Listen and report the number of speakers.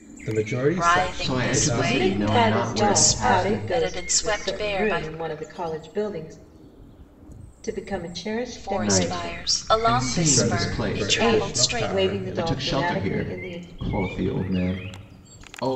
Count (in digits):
4